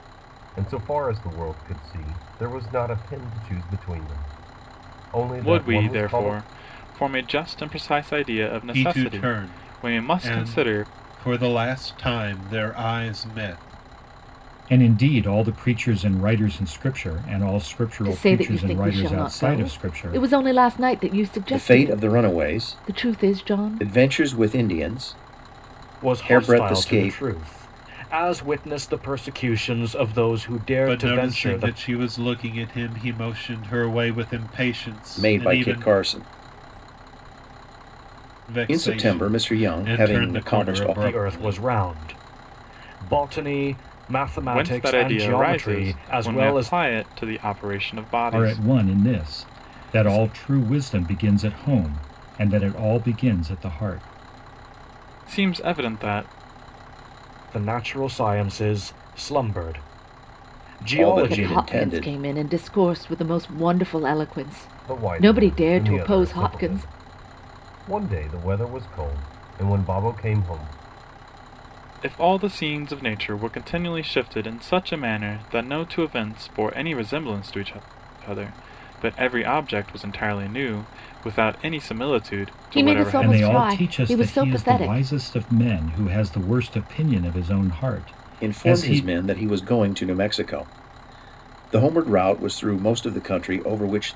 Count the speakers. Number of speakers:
7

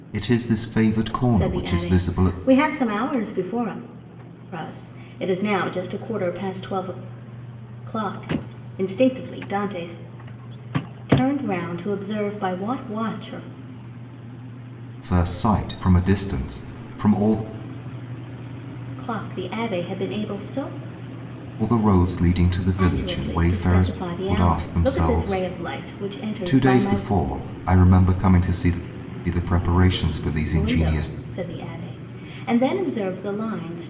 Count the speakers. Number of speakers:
2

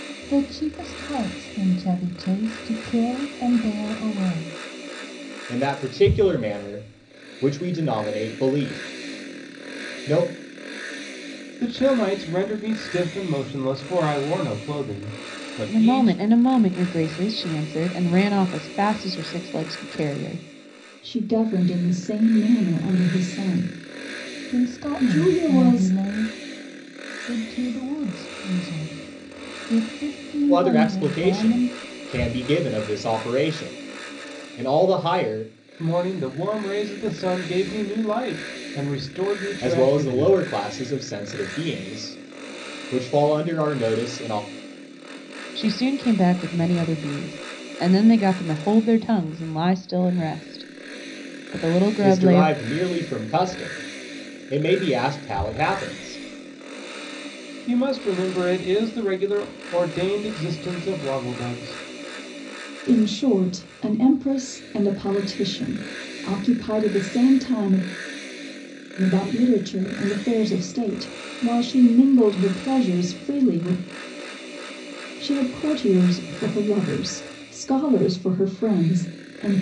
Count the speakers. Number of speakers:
5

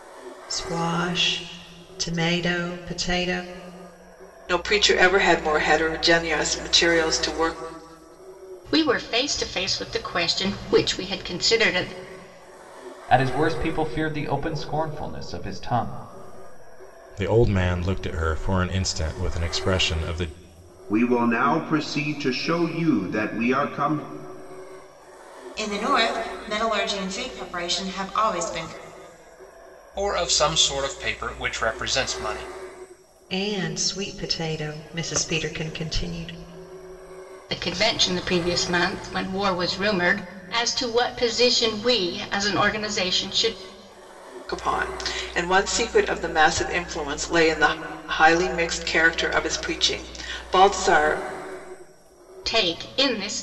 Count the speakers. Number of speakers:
8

